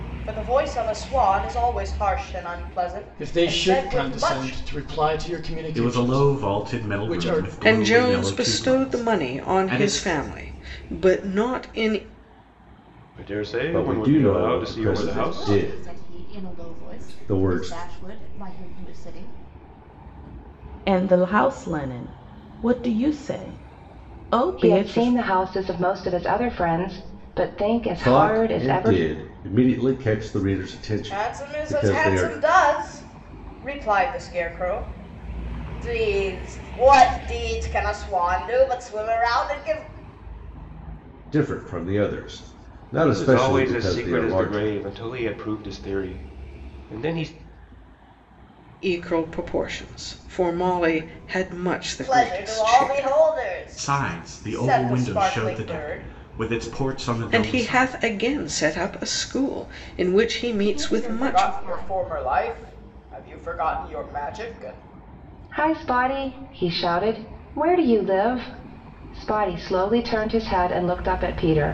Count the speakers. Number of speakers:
9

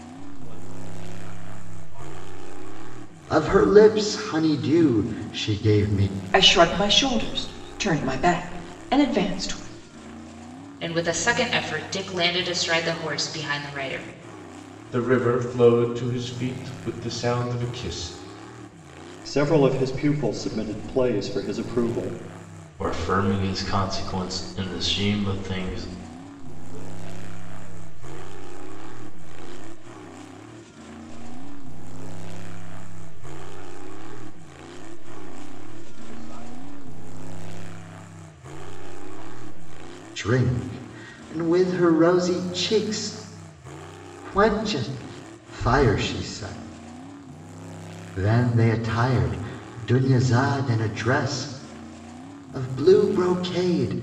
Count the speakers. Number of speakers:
7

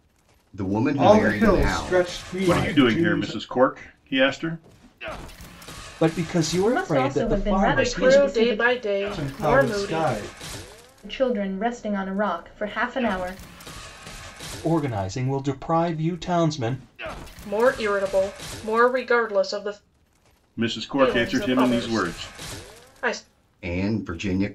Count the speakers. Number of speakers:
6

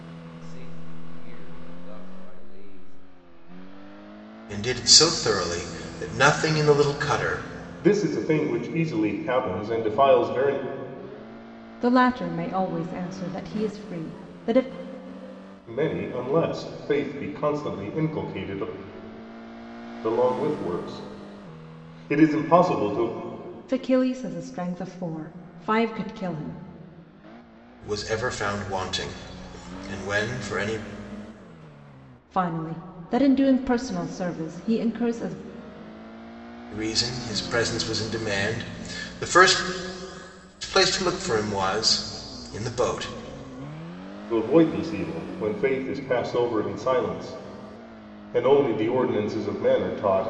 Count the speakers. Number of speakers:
4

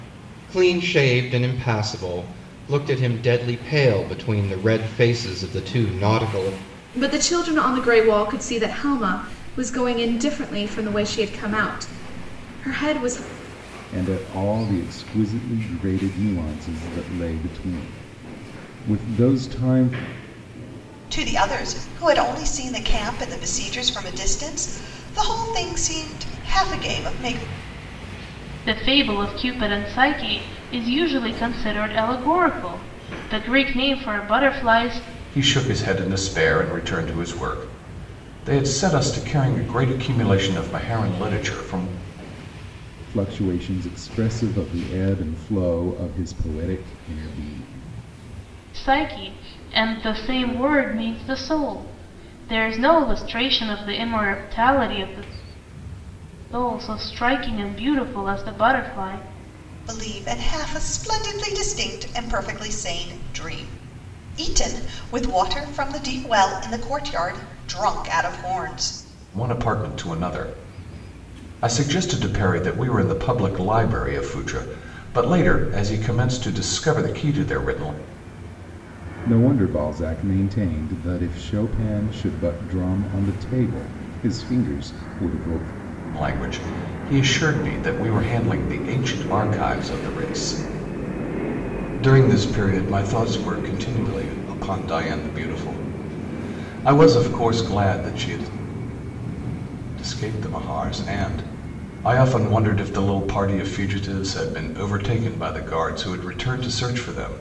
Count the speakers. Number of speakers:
6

